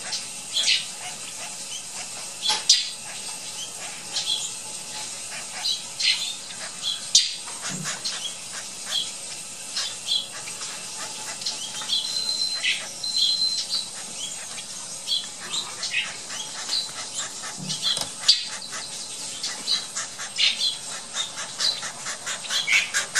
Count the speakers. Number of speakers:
zero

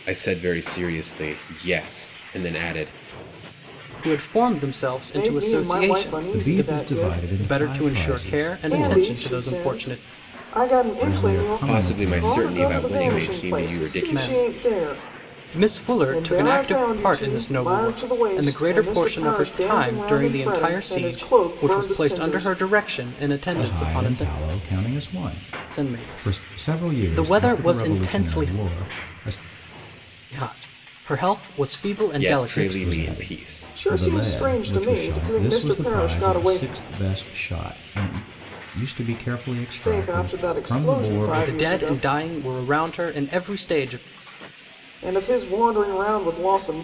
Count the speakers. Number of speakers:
four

